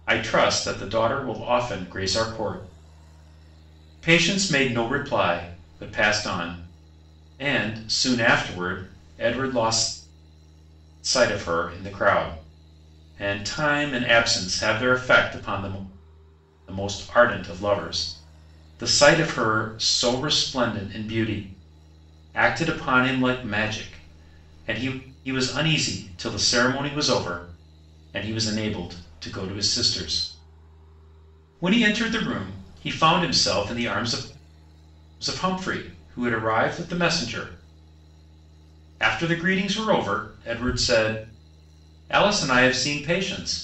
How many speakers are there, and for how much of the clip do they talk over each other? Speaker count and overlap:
1, no overlap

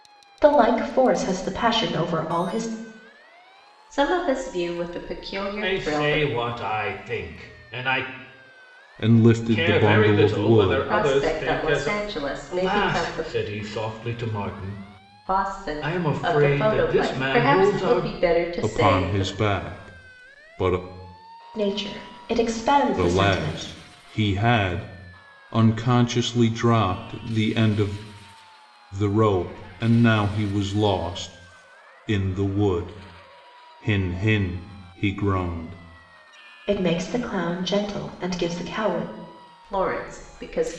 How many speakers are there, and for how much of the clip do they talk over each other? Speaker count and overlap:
4, about 19%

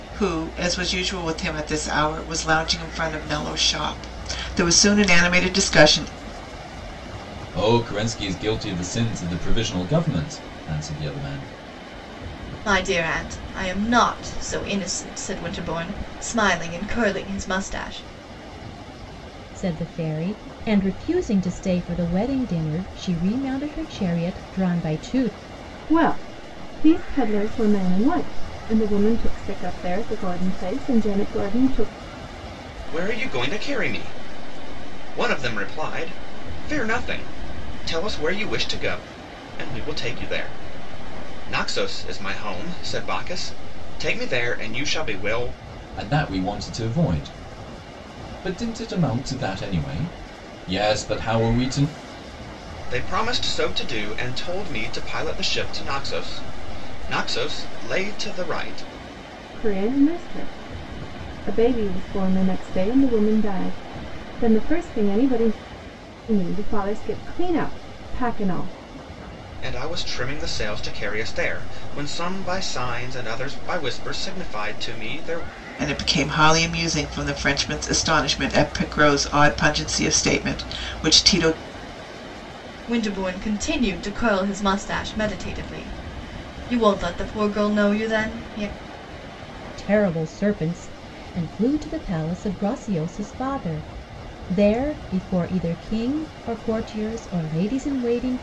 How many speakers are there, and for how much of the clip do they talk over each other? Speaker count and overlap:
6, no overlap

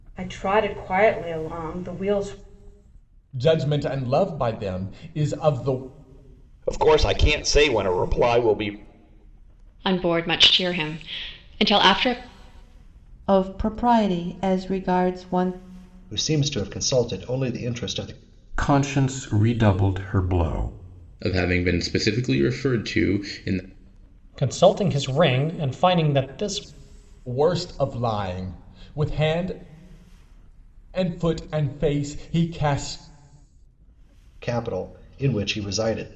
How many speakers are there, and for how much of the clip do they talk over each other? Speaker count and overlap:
9, no overlap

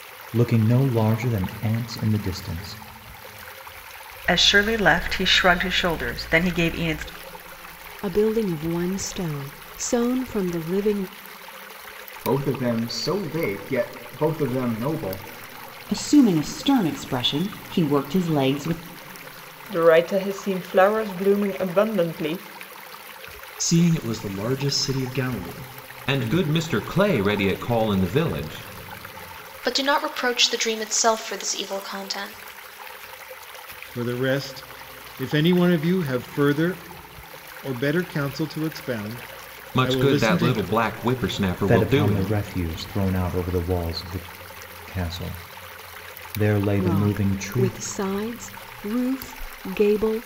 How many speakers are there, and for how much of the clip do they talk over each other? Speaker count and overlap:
10, about 6%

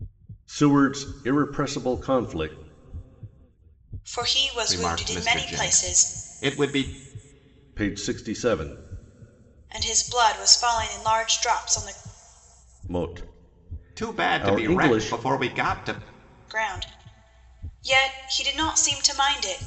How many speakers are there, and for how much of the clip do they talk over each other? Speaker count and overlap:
3, about 14%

